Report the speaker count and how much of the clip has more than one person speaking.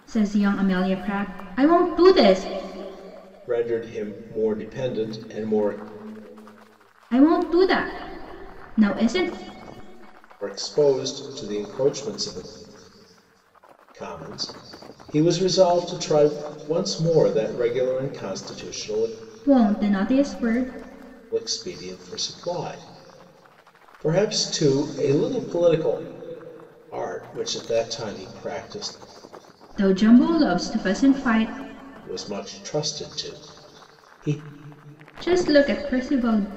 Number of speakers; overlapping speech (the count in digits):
2, no overlap